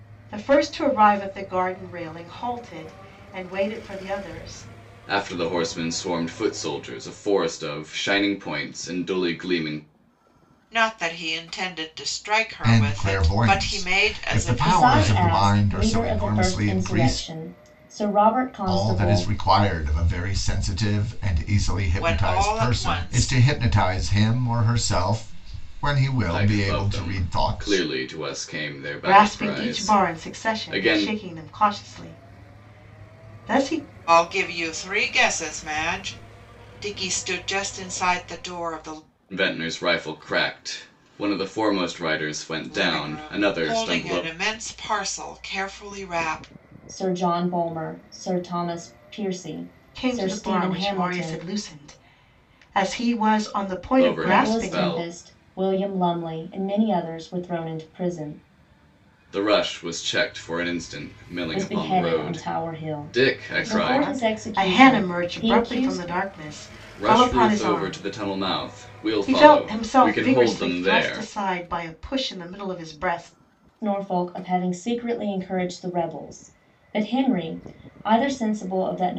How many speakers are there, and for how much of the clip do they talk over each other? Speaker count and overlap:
5, about 28%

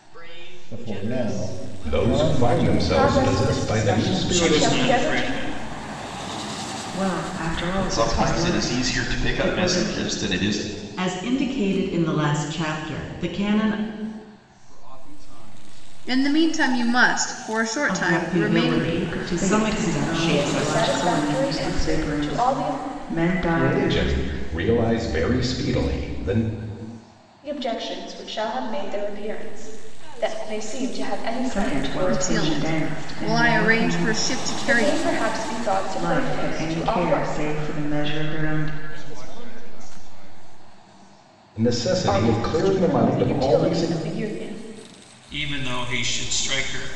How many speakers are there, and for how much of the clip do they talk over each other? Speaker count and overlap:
10, about 57%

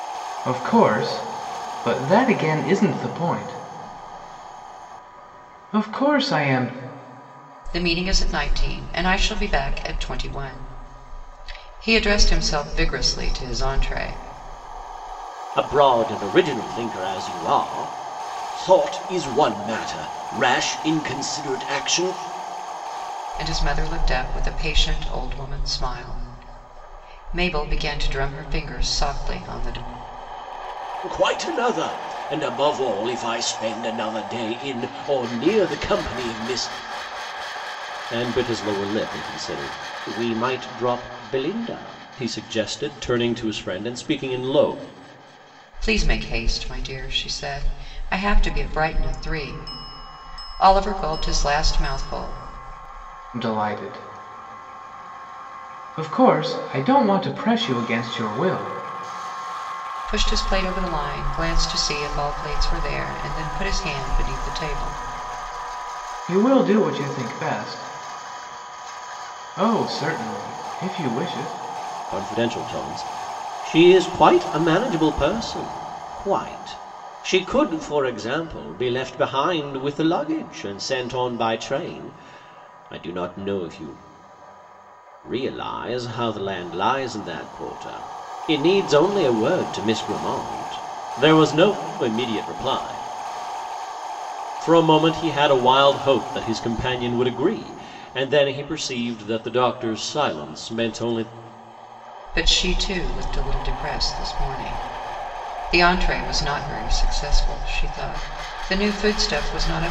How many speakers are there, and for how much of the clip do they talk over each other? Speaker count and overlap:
3, no overlap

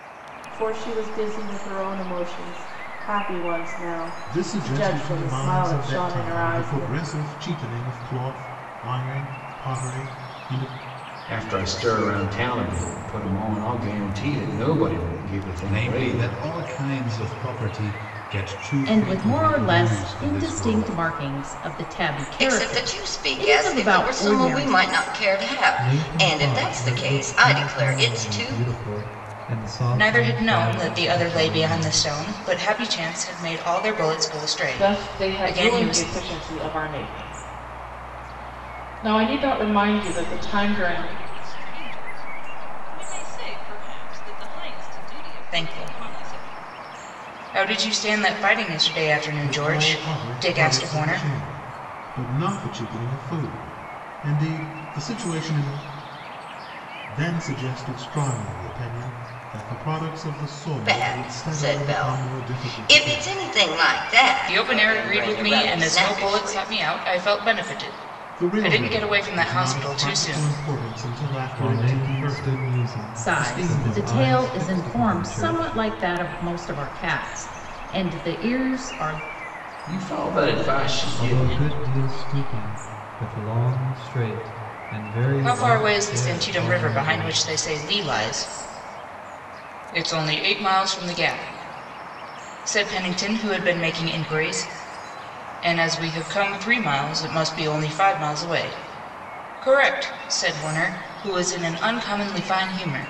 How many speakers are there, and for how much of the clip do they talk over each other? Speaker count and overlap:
10, about 33%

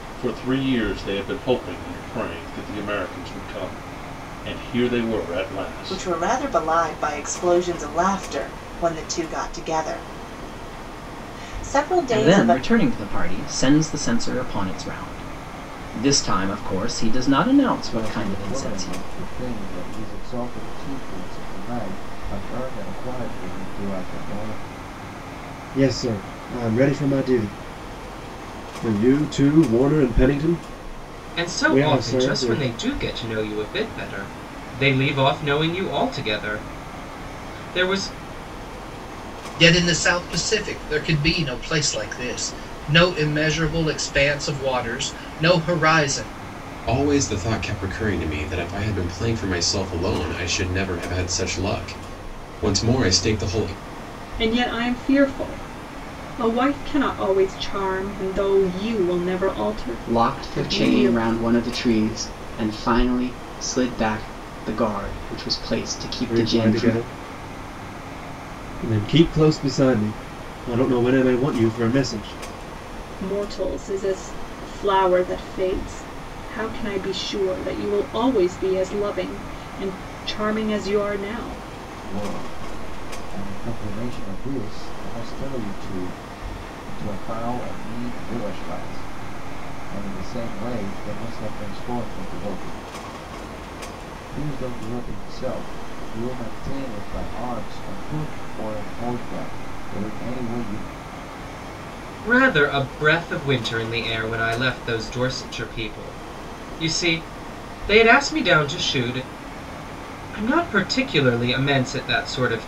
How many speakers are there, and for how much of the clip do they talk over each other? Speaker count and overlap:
10, about 5%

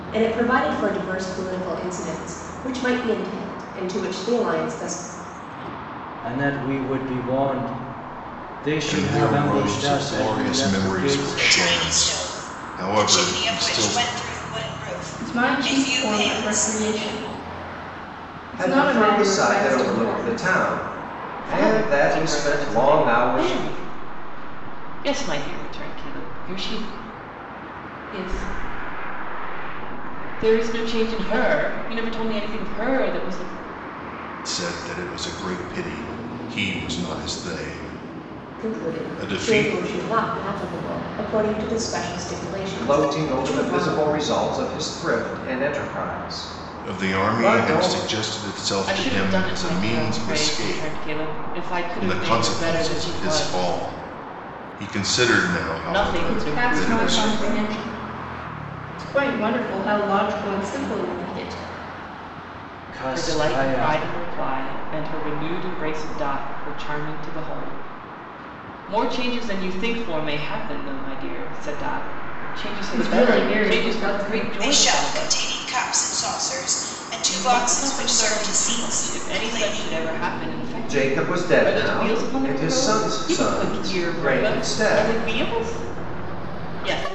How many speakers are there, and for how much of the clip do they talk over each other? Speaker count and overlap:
7, about 35%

